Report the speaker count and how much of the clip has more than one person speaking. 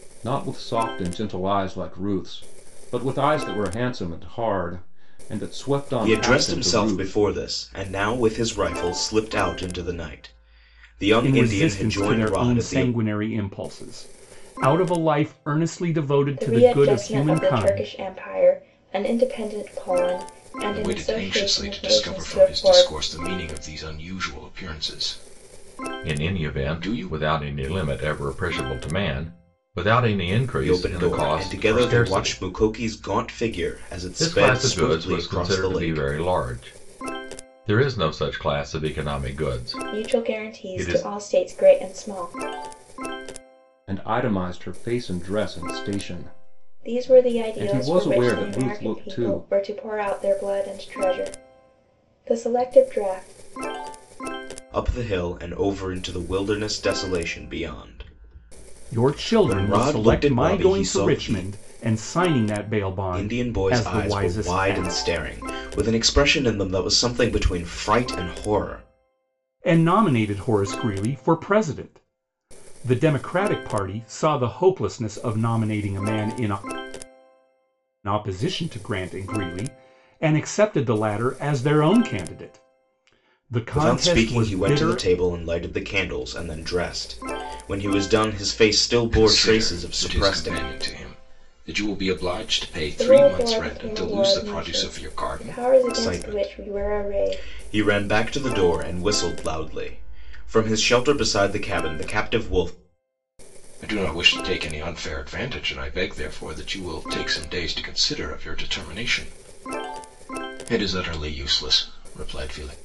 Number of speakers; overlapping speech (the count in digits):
6, about 24%